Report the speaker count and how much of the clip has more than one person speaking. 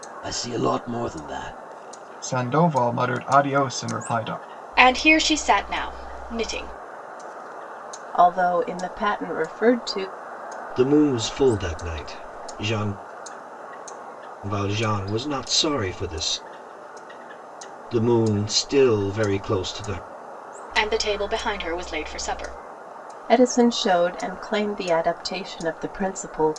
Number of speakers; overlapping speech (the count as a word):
five, no overlap